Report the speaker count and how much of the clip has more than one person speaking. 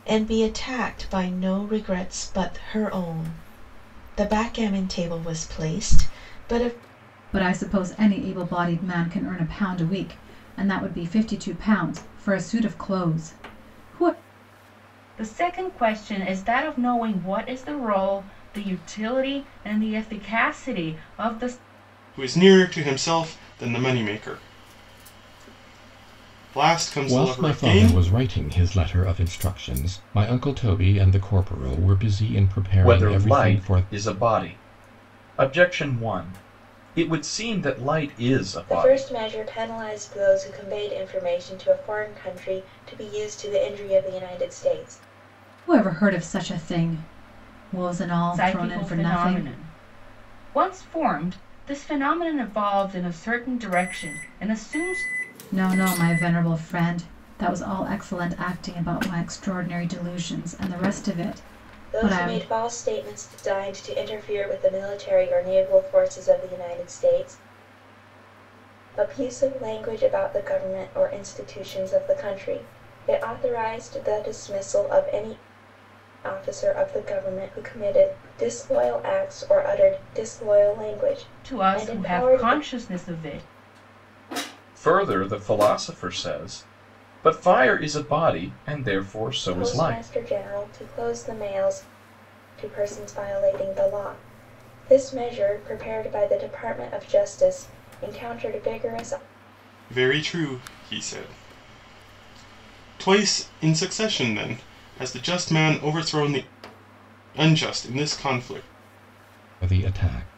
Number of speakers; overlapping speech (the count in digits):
7, about 6%